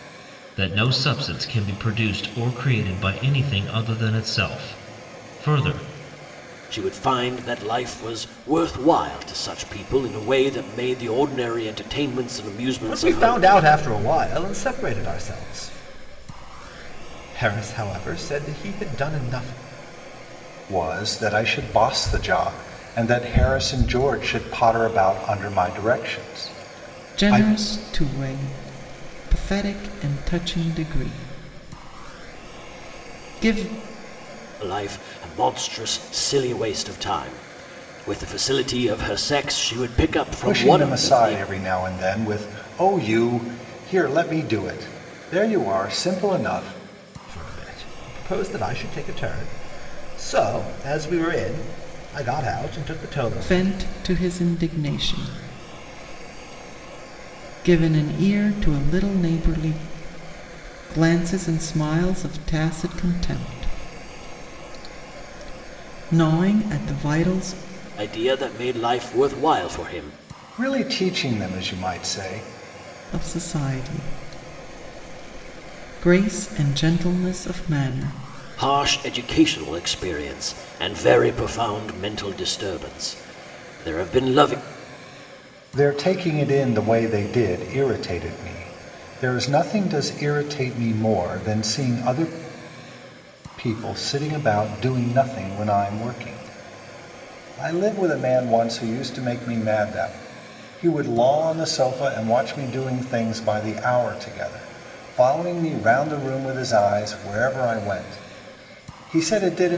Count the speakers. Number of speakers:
5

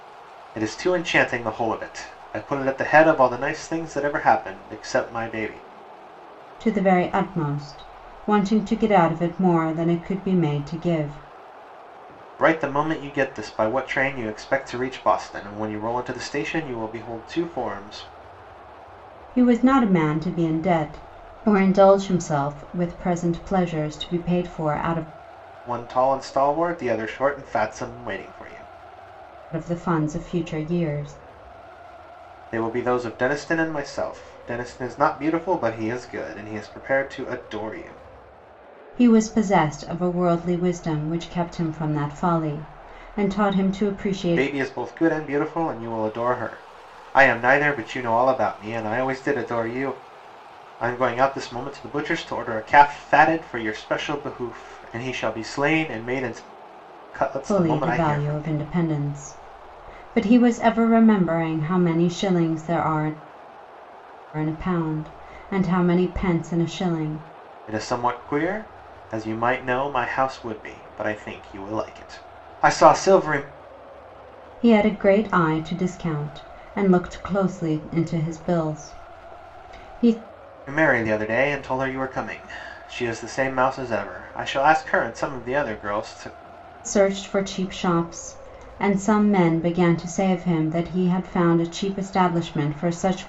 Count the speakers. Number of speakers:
2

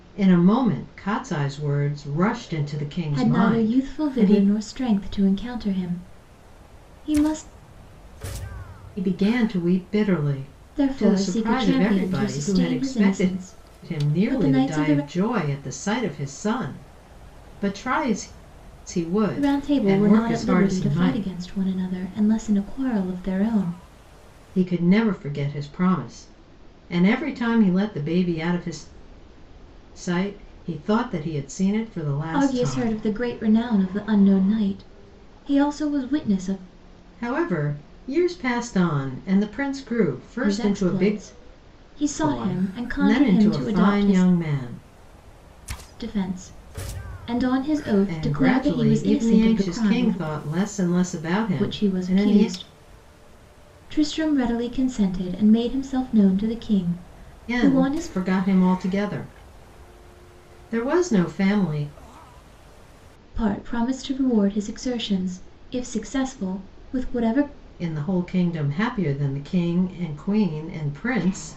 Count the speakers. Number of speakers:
2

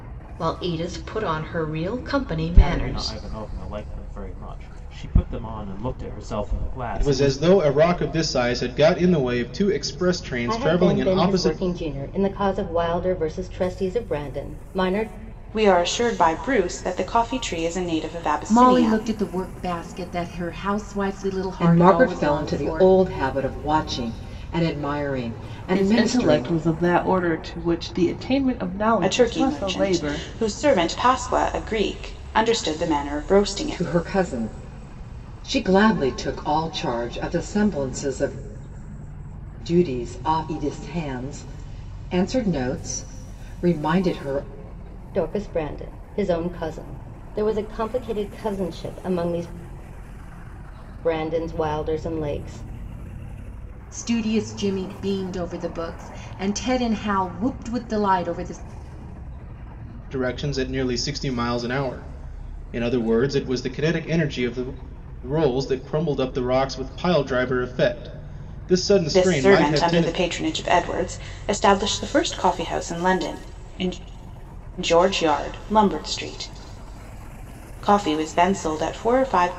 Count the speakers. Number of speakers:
8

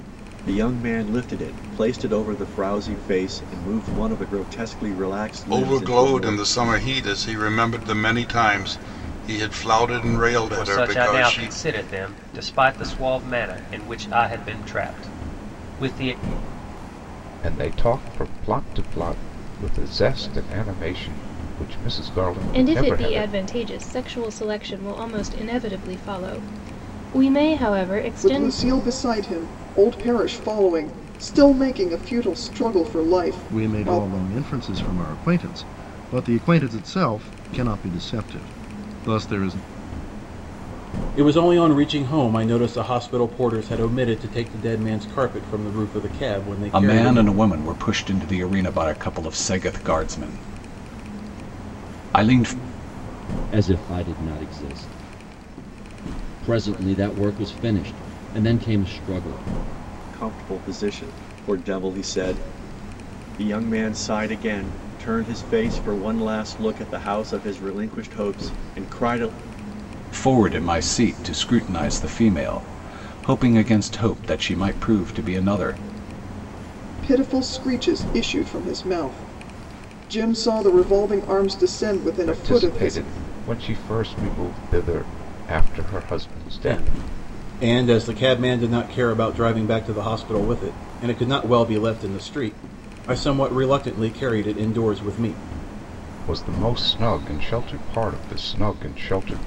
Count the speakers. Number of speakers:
10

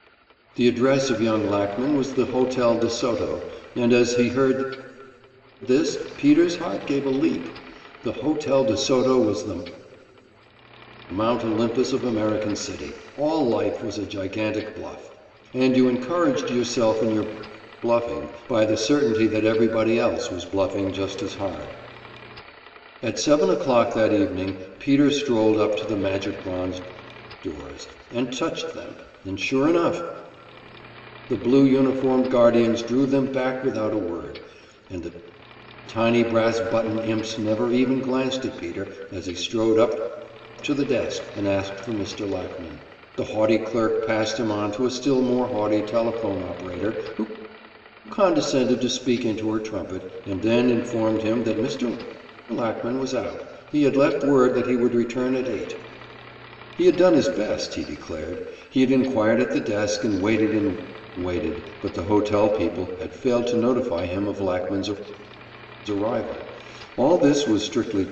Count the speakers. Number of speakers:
1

